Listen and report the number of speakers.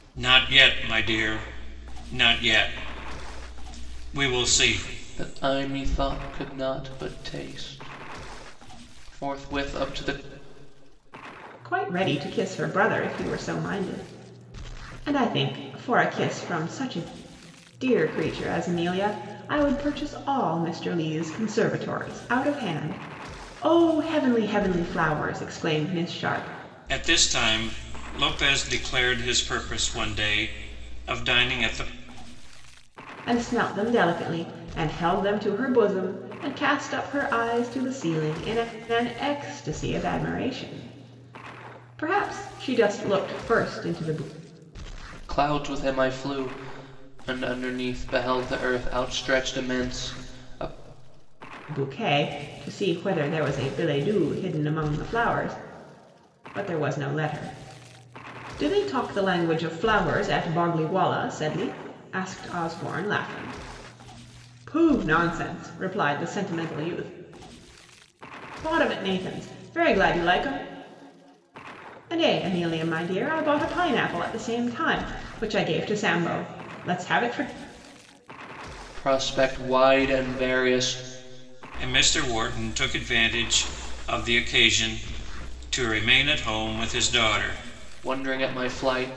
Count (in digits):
3